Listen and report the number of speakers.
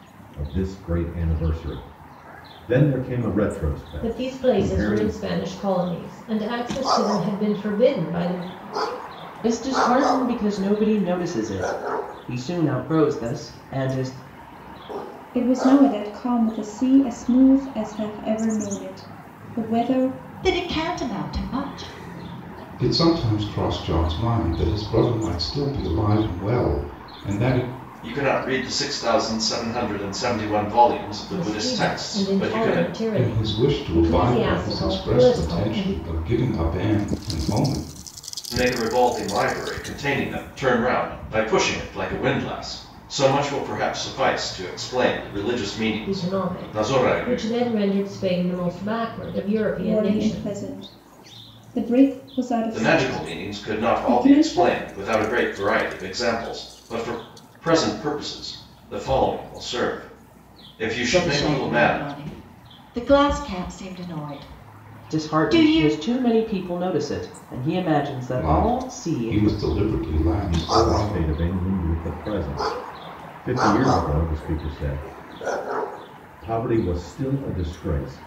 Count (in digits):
7